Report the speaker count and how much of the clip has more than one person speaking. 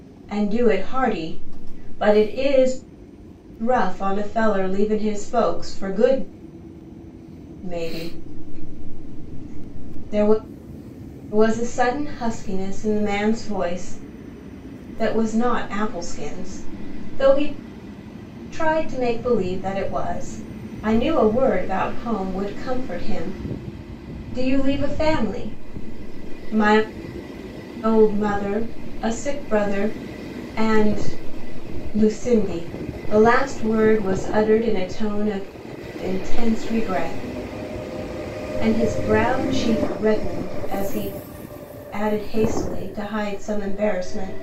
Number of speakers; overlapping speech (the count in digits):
1, no overlap